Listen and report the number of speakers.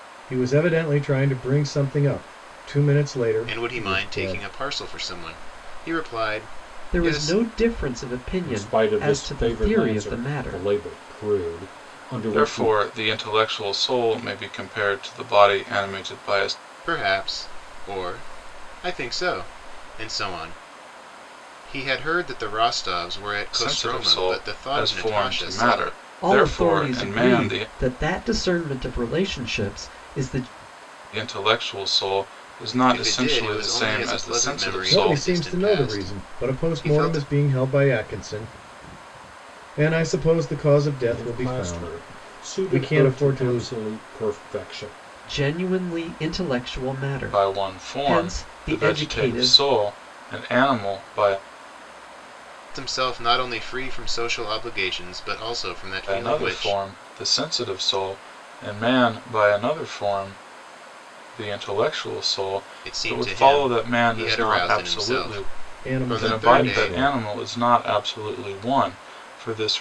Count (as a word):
five